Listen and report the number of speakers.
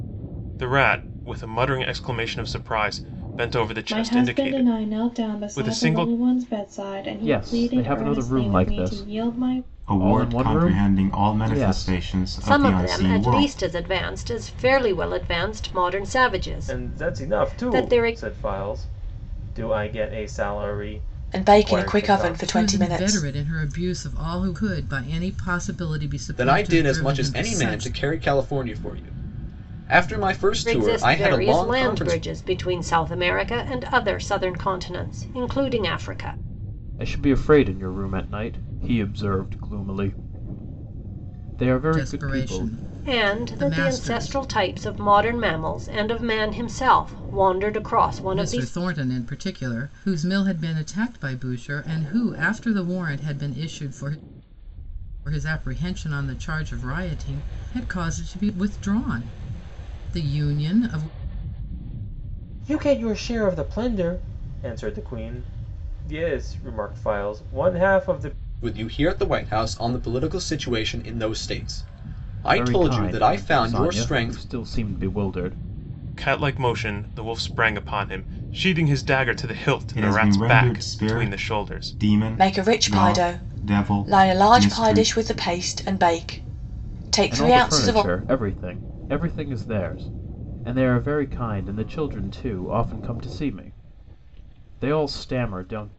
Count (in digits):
9